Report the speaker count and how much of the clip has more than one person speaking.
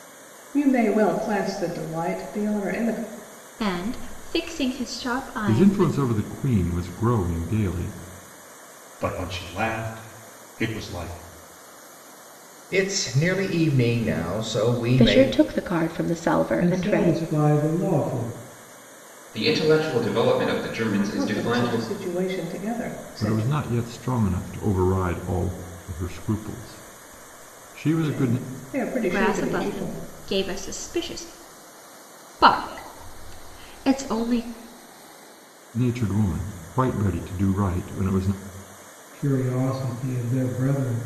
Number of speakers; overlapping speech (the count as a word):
eight, about 10%